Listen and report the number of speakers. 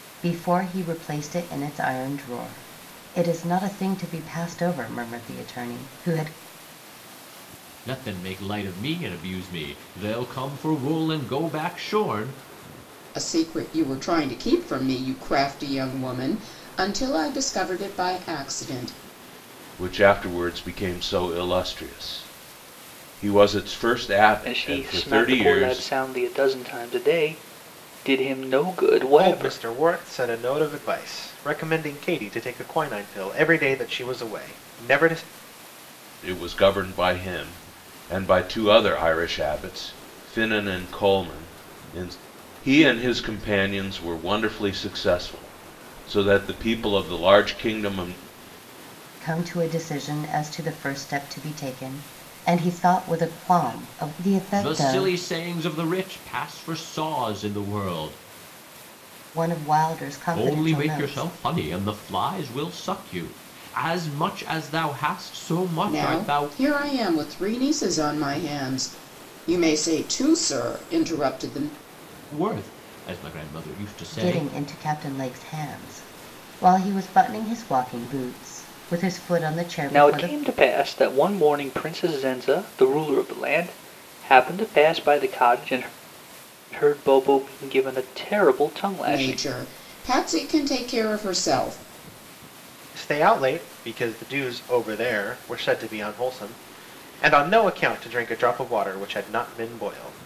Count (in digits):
6